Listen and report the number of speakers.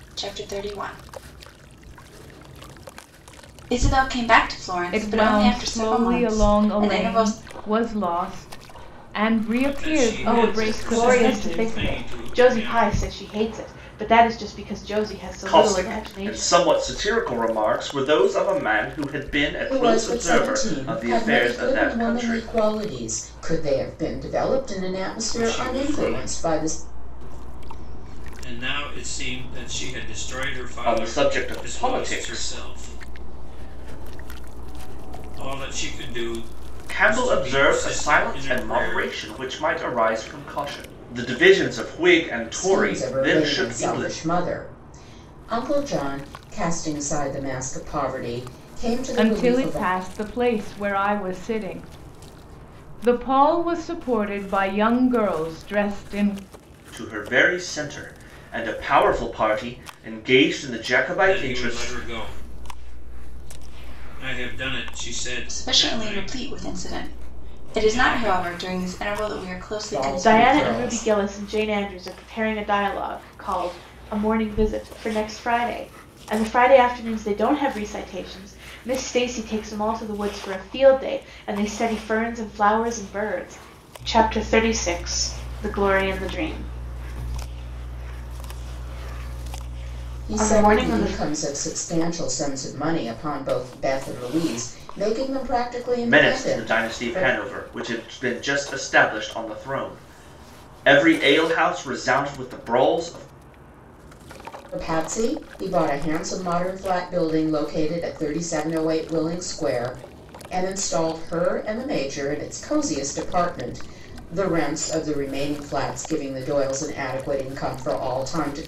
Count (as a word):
six